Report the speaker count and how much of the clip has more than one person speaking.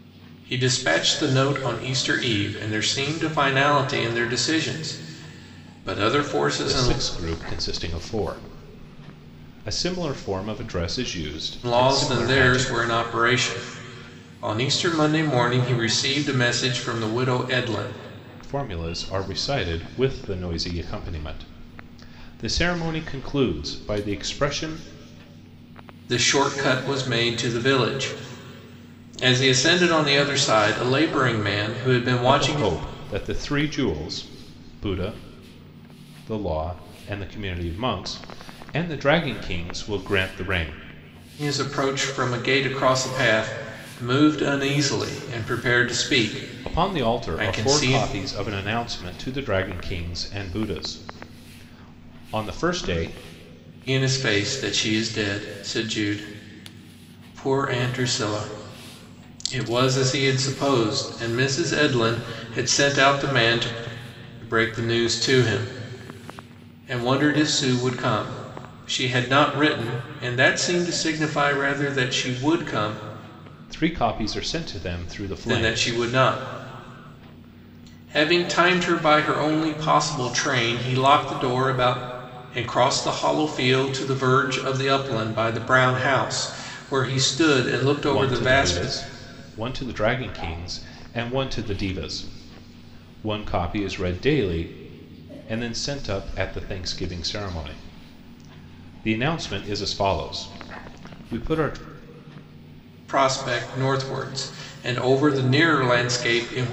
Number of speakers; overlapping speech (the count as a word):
two, about 4%